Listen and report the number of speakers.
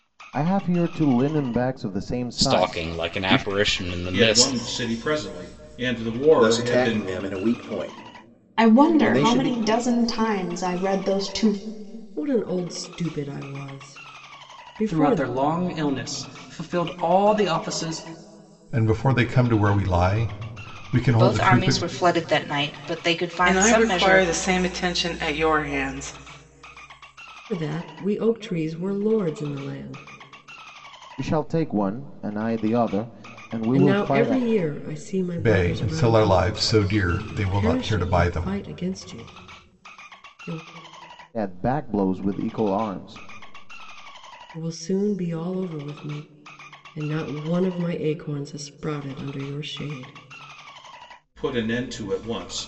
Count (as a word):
ten